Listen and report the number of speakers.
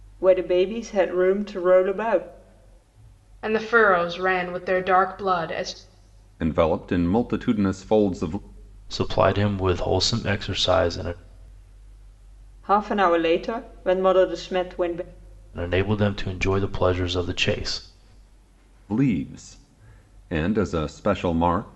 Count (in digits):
4